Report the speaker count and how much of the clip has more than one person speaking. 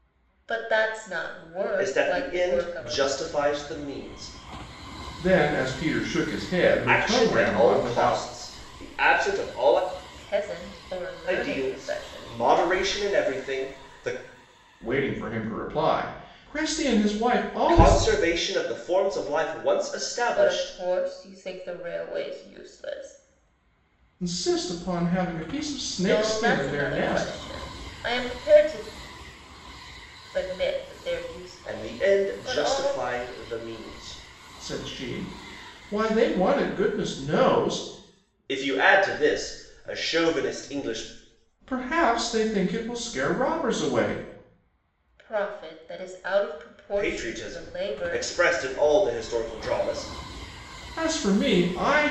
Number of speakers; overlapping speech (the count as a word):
three, about 17%